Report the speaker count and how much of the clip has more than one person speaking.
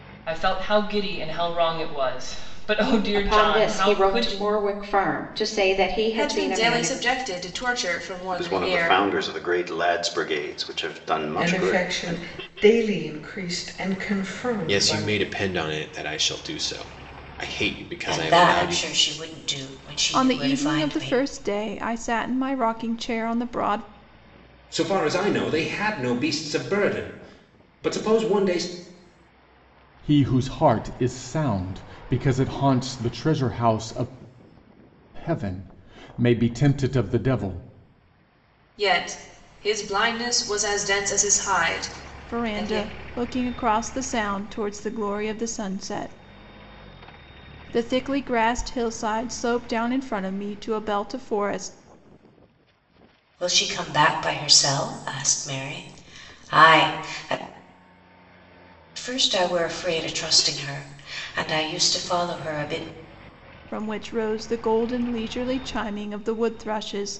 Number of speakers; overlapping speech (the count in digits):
10, about 10%